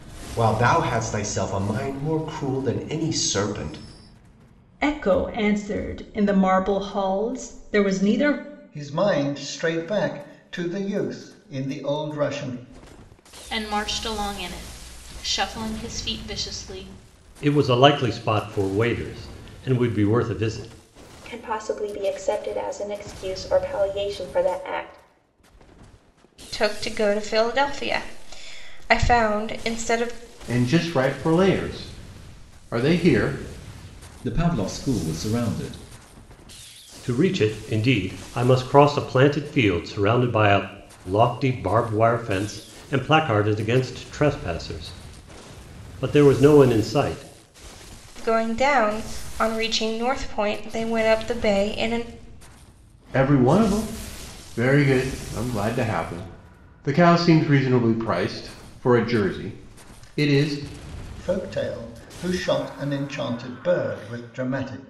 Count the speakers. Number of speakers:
nine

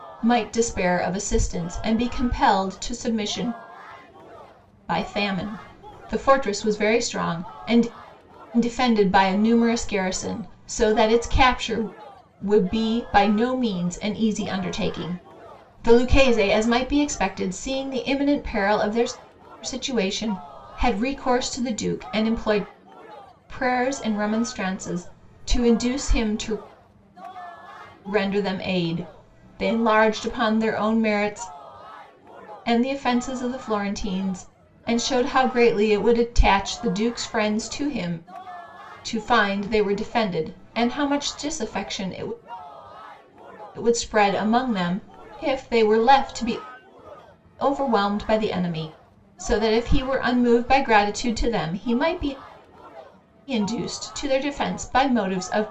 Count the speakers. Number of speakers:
one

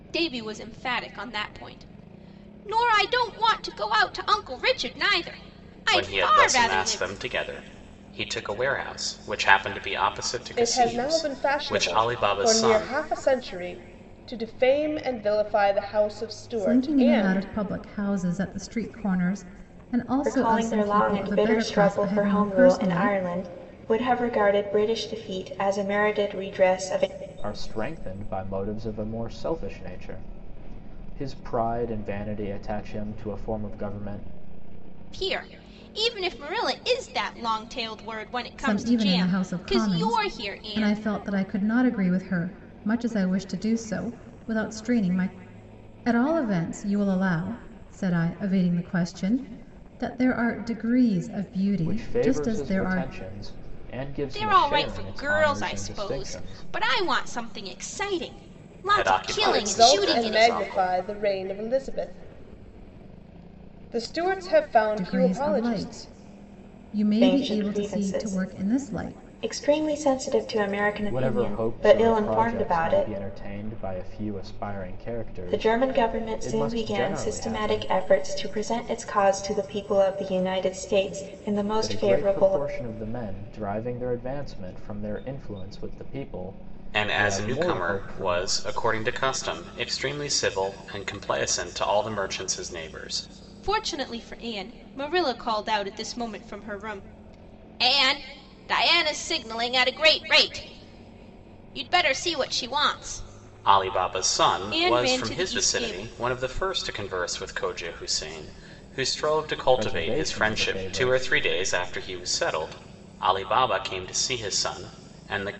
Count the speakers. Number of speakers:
six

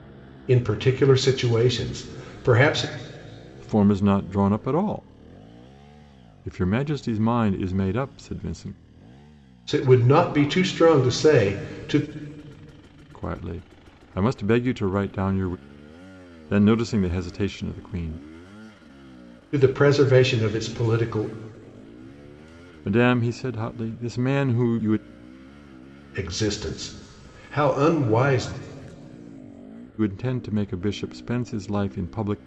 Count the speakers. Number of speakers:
two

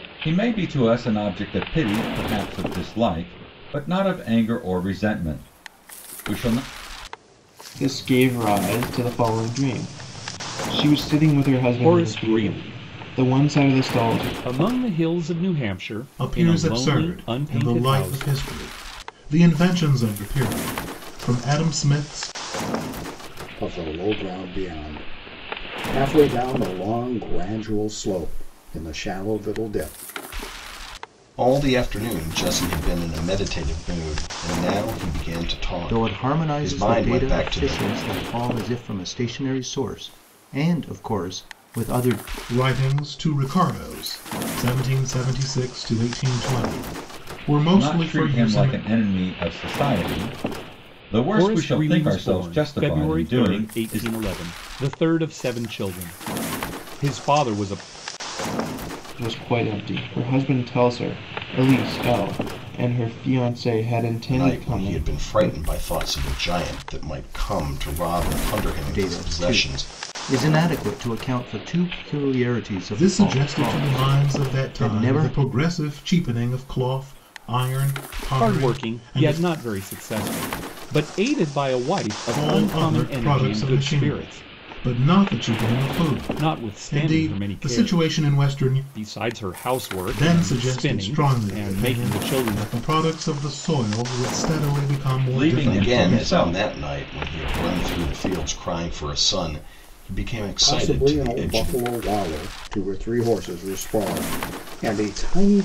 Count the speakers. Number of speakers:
seven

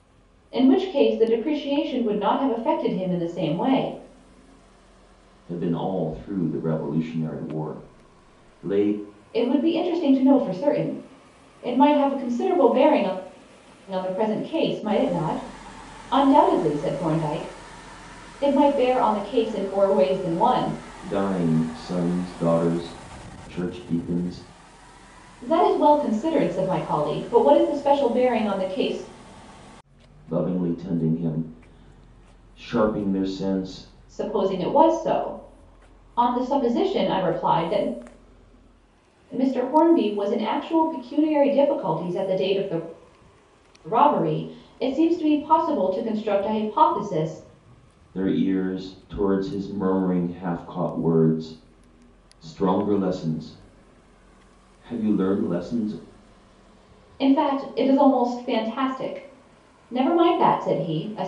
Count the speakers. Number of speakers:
two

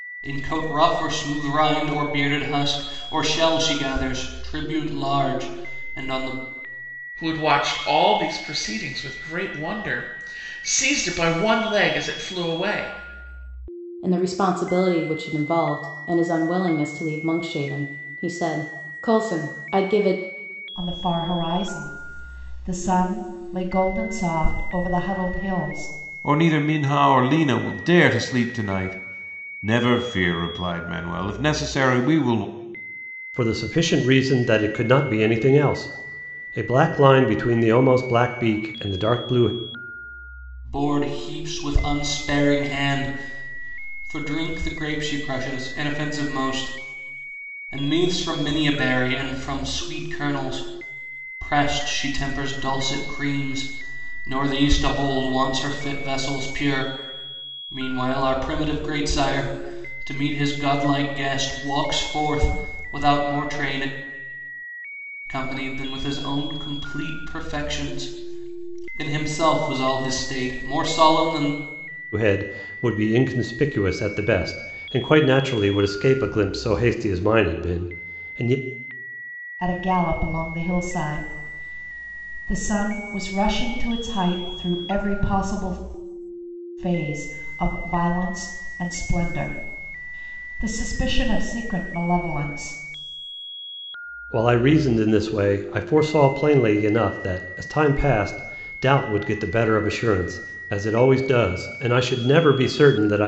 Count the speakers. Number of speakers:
six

